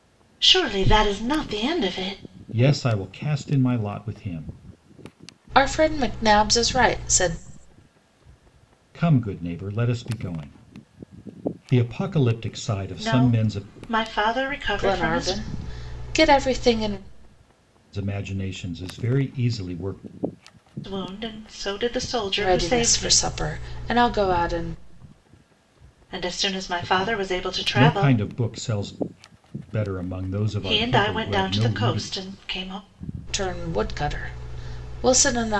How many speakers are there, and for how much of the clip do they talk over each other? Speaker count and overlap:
three, about 14%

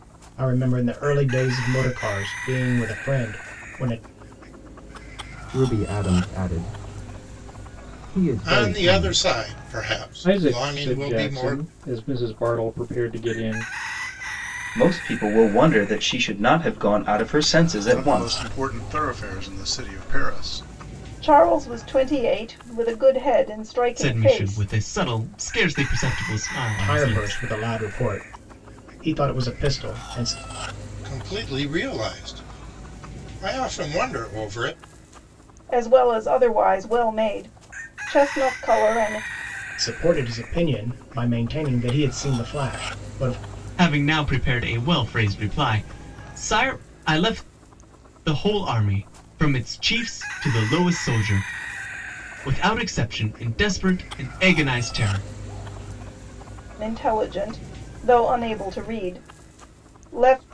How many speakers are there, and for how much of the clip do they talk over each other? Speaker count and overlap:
eight, about 7%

